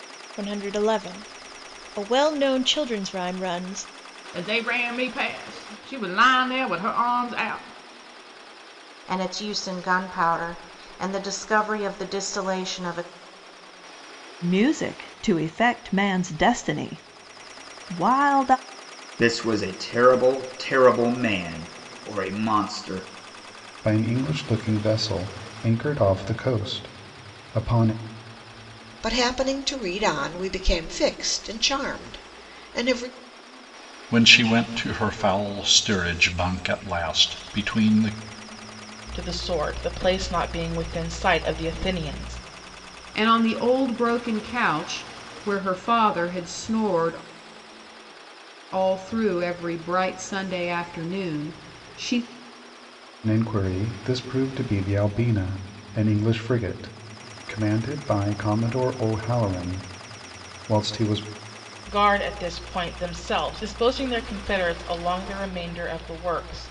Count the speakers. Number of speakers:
ten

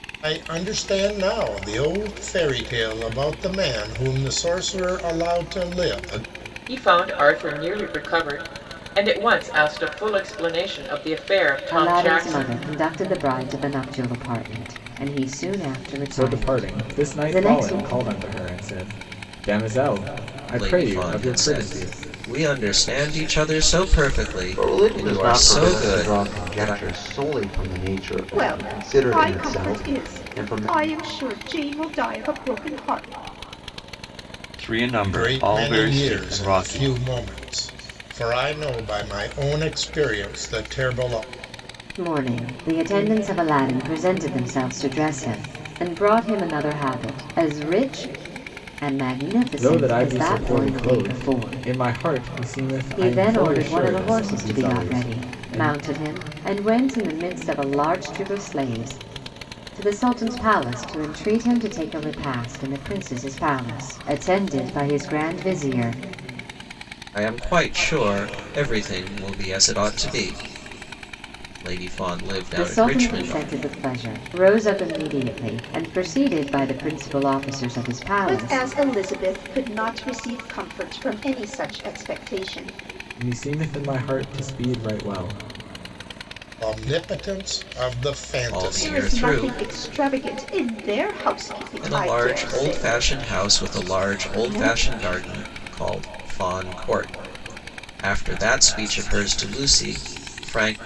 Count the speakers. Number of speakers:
eight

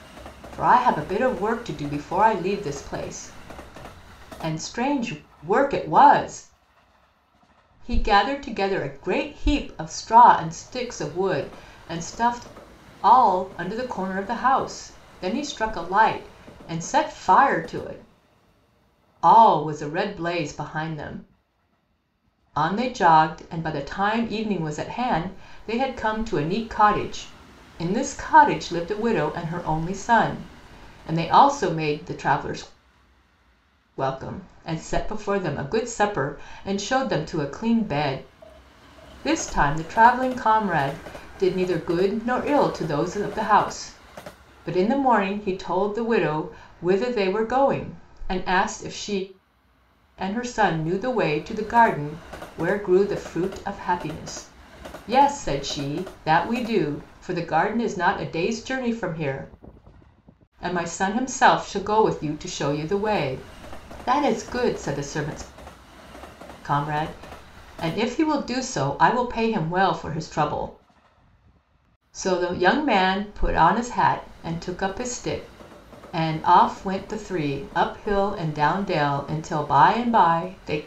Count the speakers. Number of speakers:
one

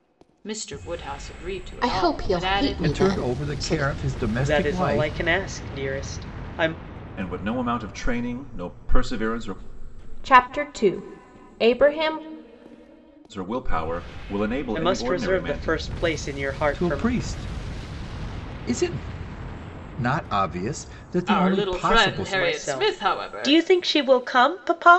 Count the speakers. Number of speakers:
six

